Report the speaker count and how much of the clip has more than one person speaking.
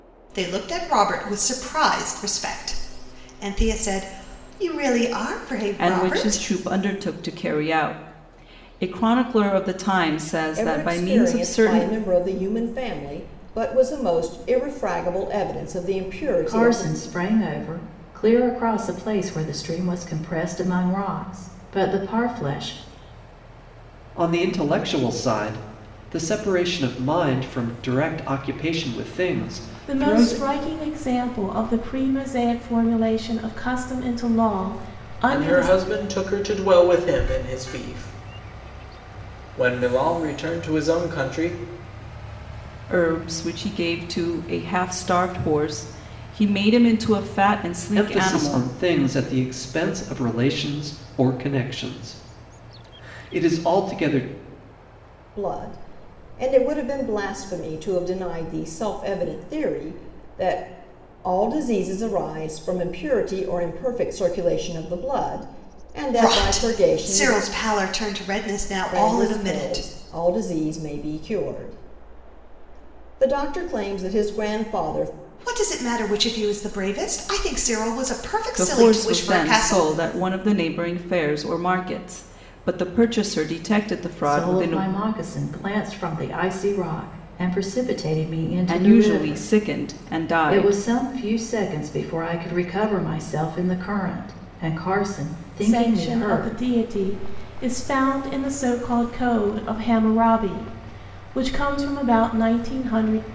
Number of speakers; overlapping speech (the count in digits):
7, about 11%